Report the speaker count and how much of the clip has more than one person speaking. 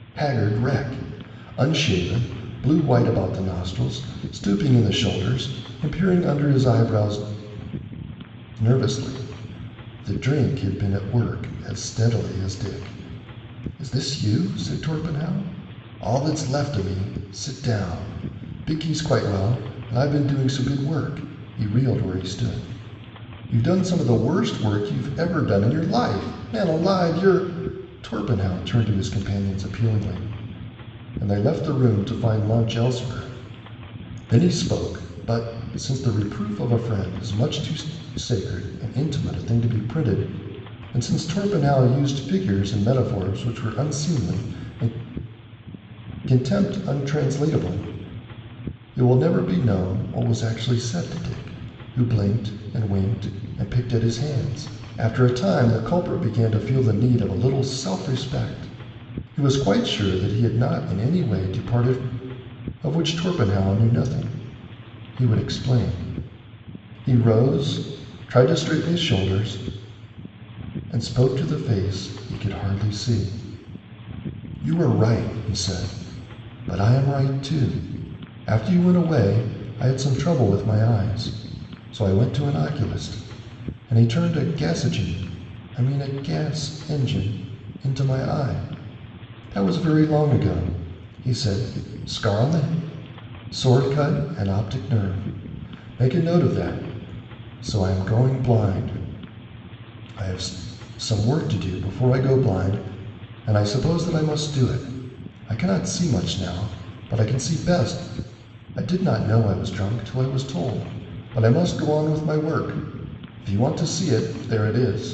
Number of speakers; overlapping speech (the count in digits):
1, no overlap